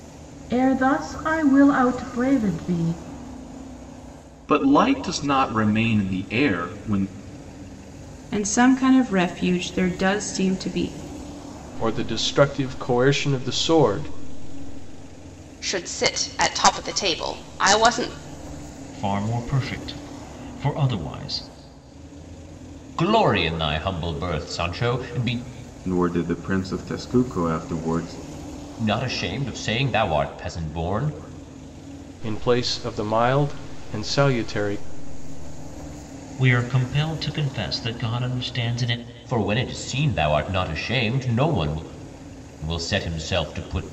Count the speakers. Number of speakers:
8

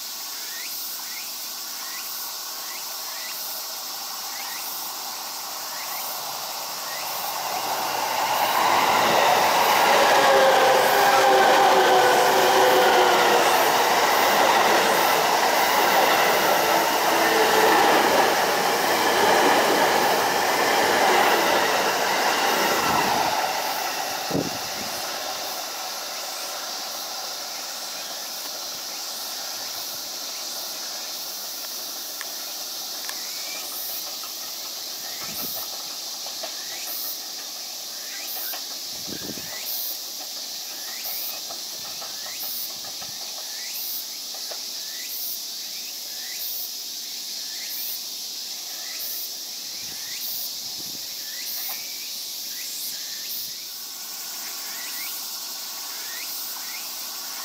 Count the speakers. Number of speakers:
0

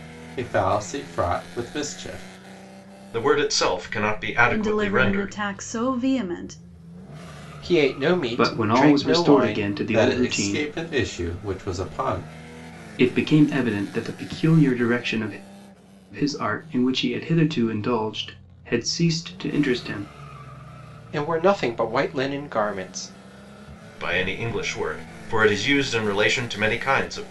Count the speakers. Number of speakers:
5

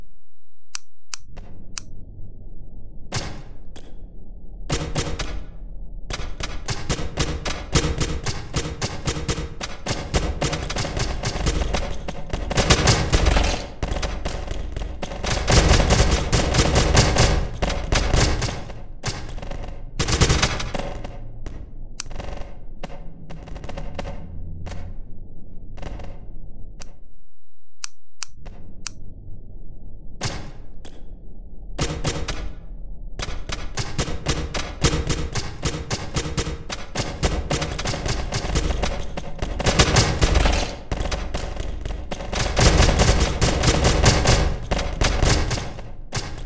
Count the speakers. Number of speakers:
0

